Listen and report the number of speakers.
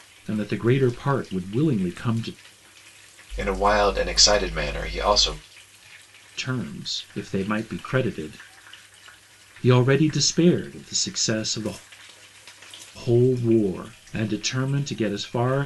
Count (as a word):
two